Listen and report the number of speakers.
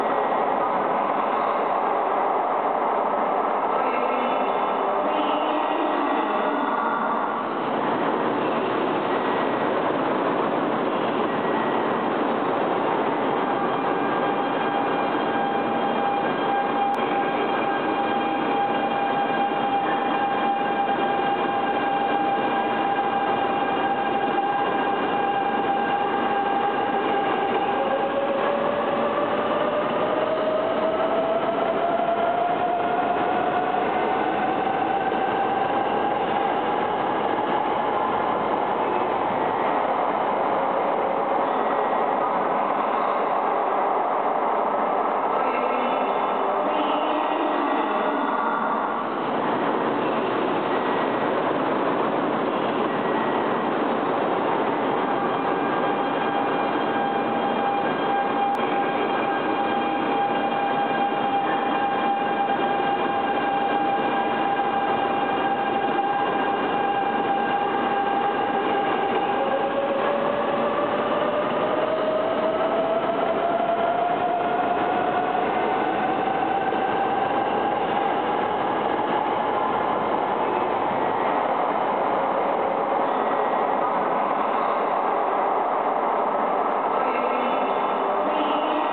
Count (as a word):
zero